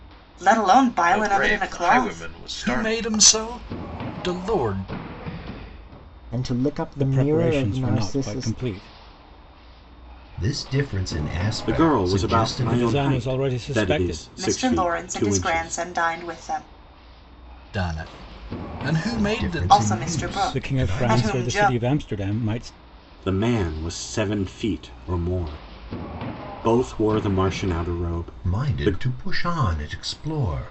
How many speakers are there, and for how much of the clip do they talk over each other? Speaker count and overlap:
seven, about 35%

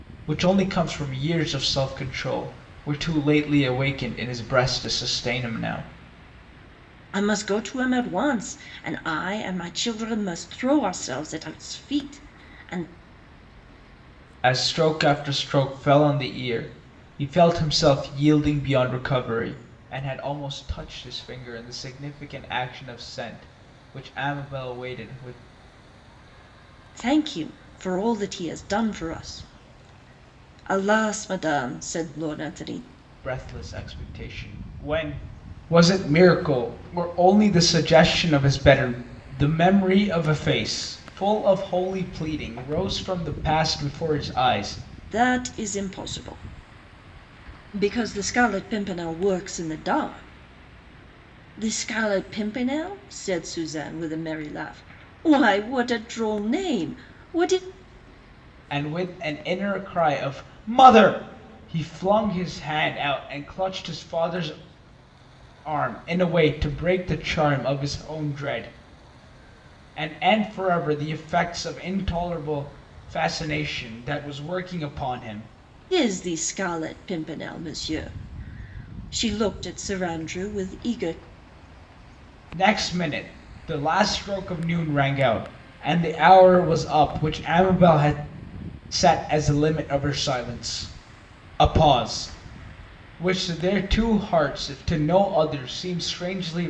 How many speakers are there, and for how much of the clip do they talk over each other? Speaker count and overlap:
two, no overlap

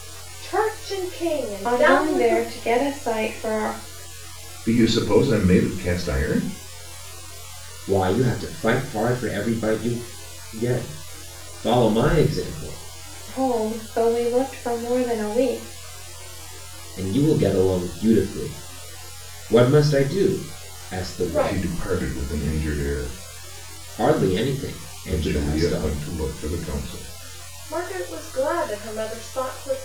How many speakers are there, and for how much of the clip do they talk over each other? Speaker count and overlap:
four, about 8%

